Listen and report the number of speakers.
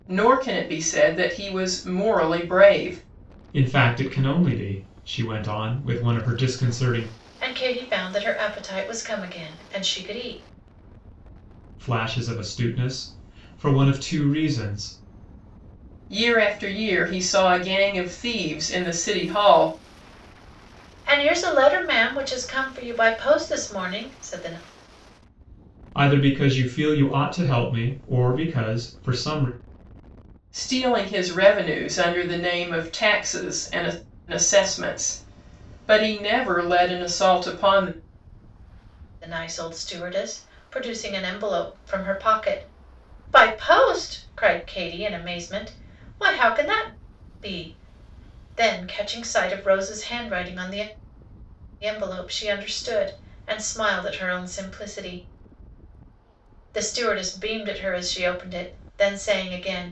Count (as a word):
three